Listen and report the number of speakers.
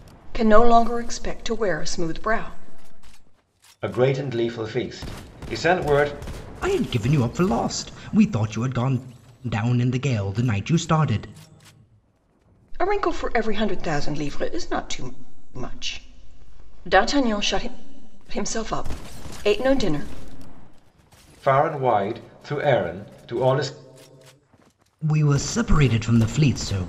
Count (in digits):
3